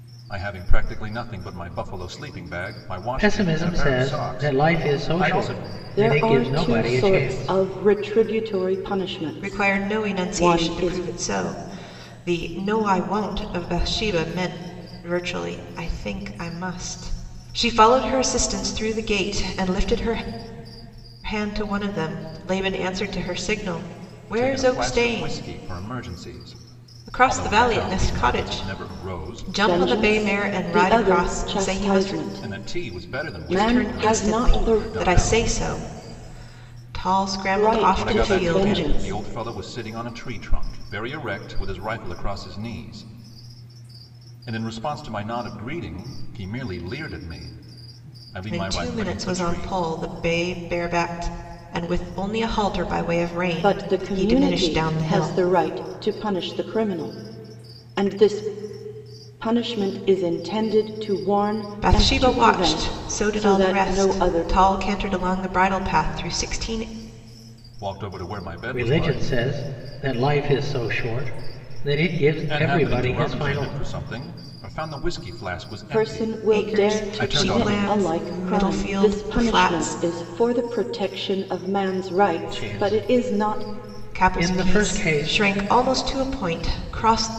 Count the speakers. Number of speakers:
4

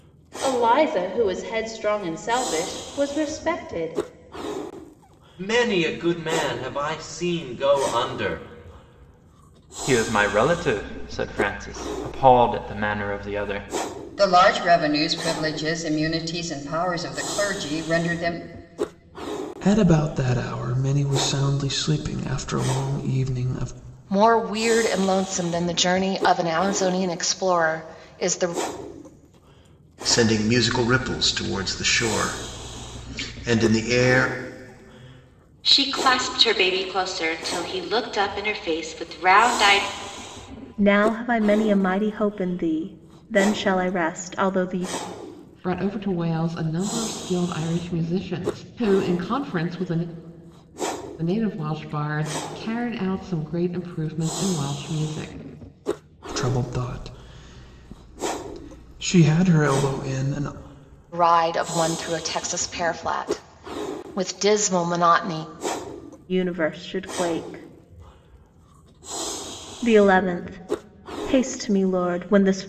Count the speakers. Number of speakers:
10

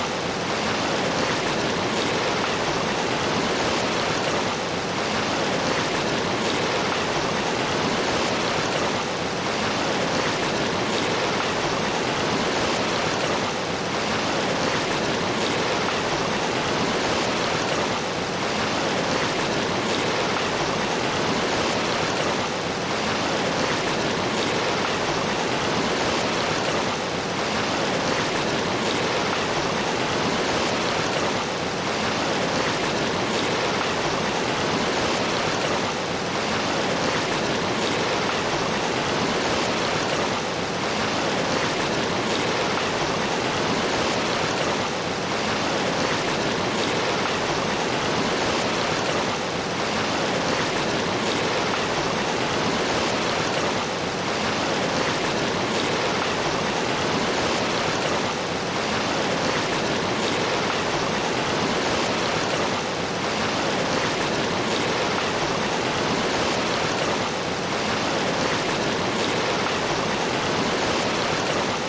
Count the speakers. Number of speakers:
0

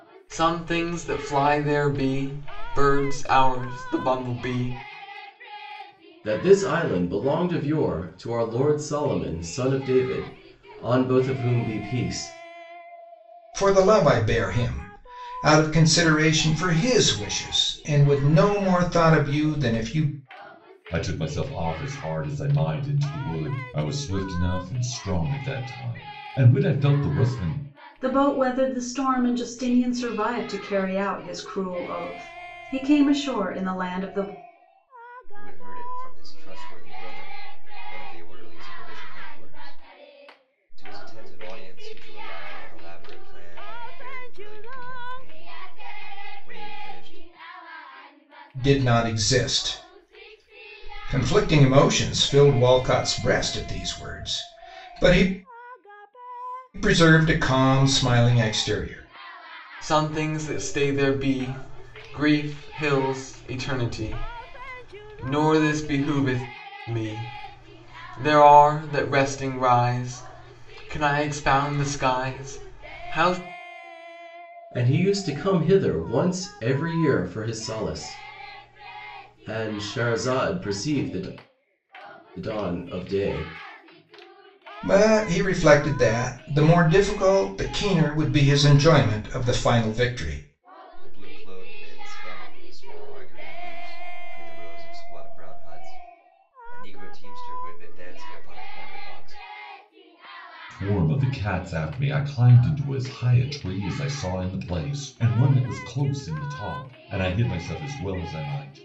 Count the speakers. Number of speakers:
6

